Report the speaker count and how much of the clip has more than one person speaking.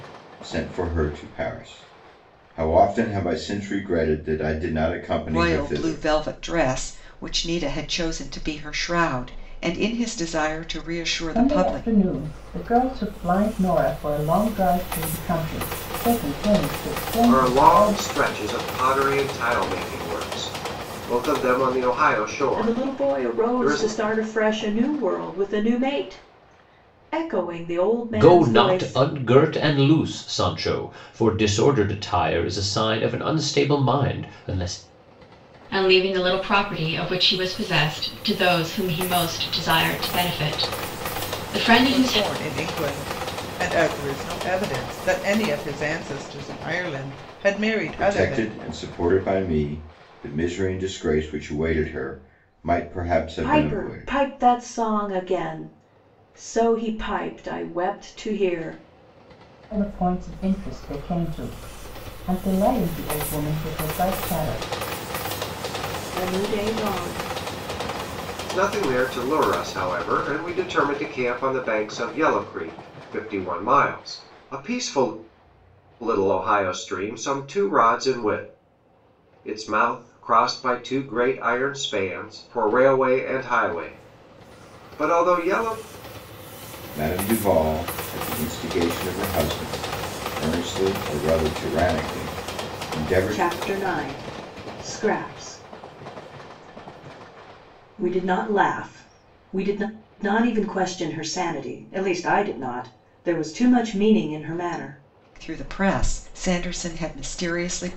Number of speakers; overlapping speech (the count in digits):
8, about 6%